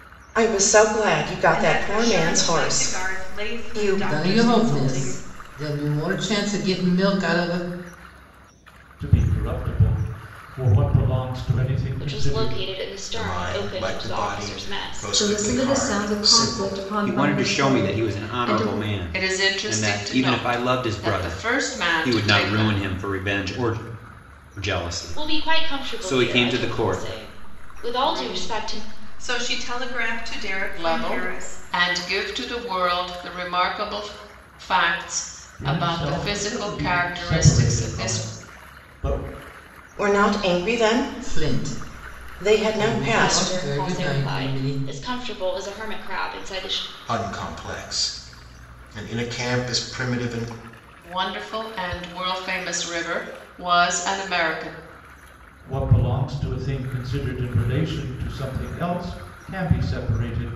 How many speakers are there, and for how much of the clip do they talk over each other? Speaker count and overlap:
9, about 39%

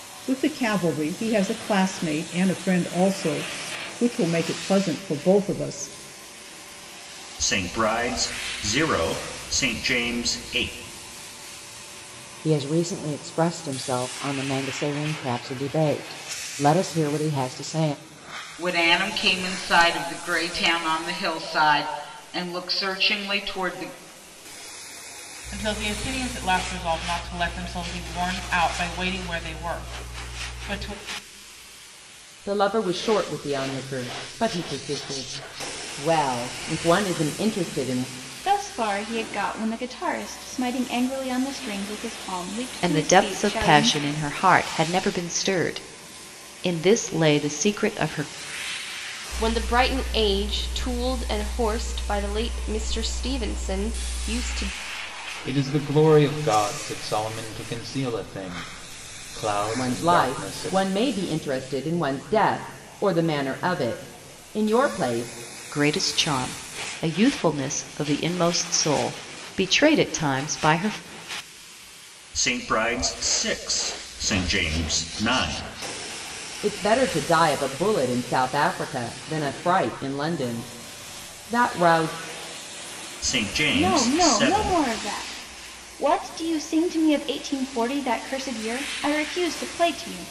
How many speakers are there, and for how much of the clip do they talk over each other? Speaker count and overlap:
10, about 4%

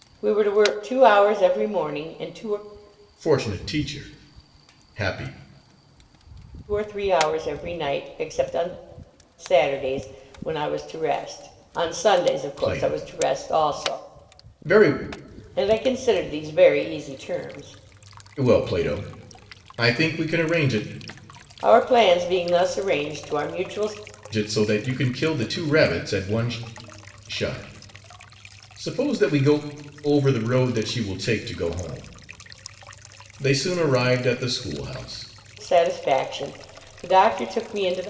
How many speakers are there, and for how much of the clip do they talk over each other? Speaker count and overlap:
2, about 4%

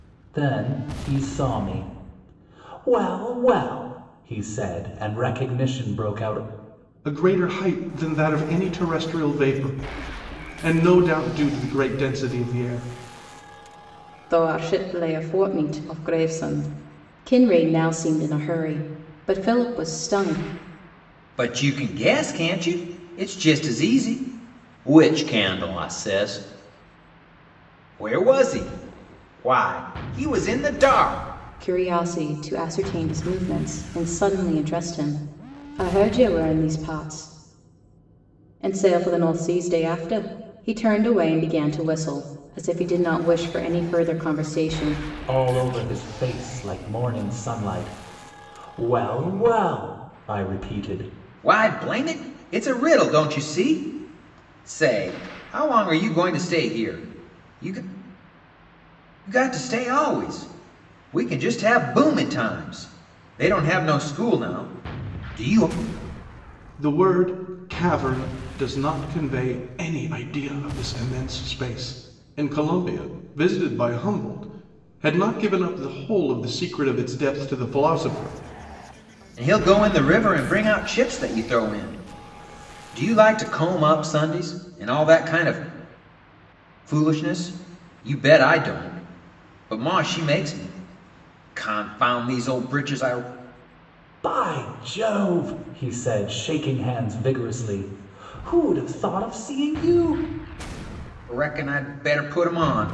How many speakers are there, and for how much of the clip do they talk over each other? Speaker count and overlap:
4, no overlap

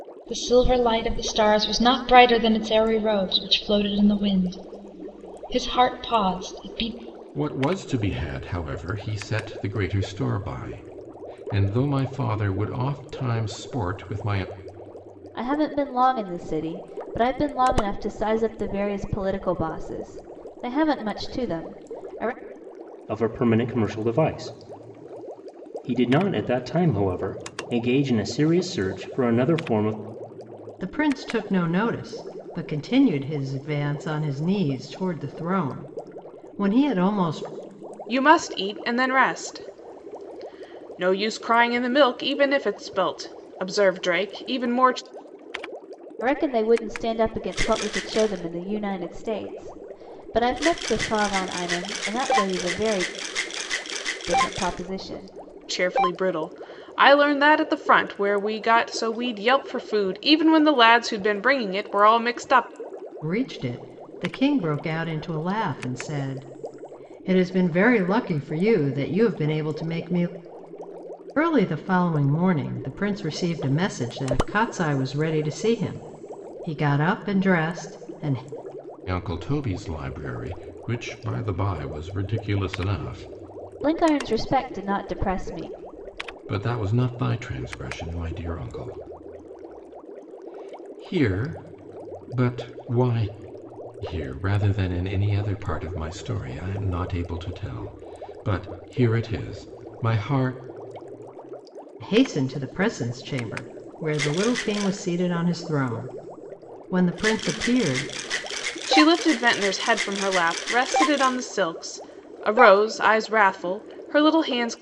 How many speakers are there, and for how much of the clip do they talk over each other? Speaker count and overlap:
6, no overlap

